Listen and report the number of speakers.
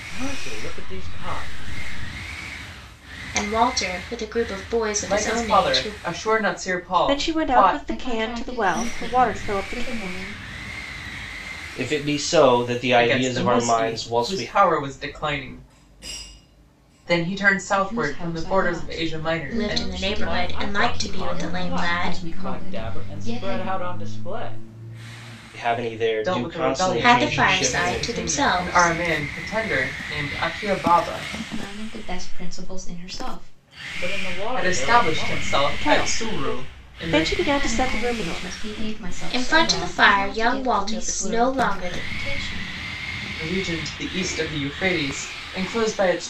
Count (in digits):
6